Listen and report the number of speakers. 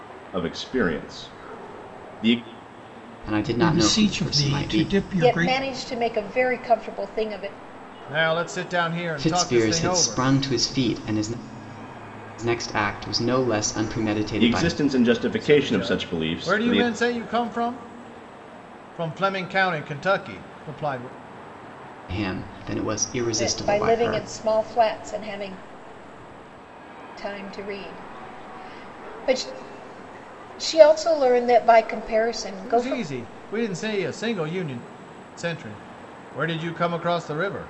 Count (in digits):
5